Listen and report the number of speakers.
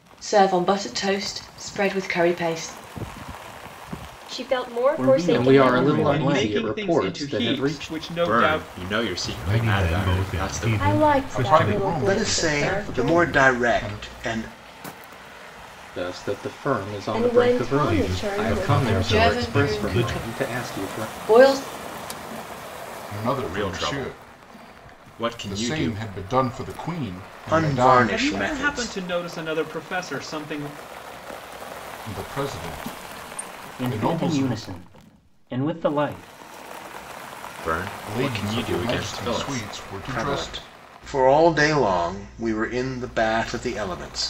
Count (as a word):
ten